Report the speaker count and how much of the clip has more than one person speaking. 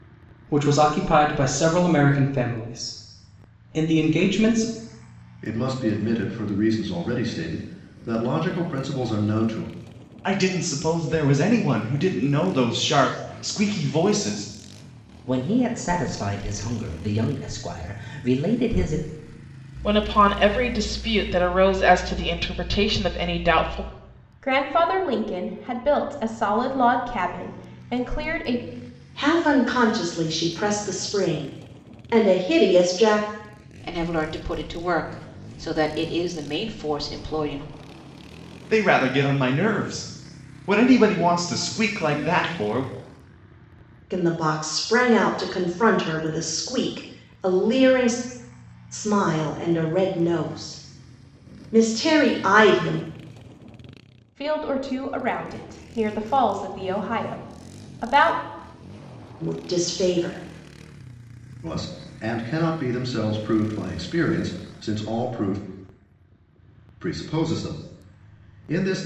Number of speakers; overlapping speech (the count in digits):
8, no overlap